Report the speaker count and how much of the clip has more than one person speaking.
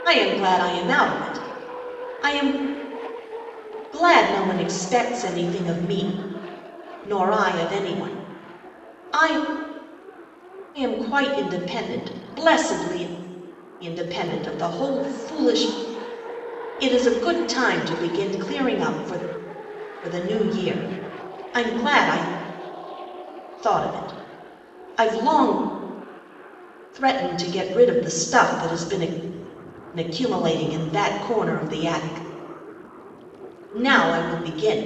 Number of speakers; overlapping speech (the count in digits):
1, no overlap